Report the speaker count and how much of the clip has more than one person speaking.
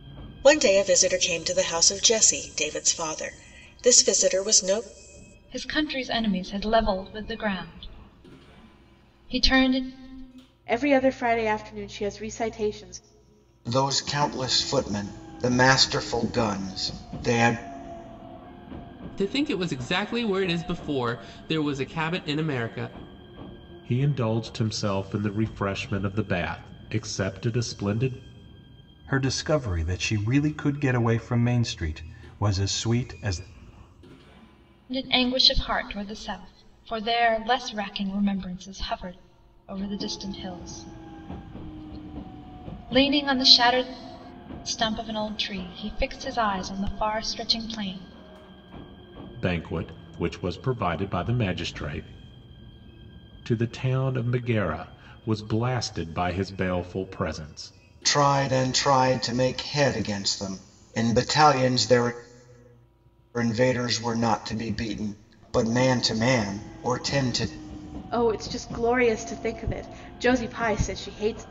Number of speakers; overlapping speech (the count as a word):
seven, no overlap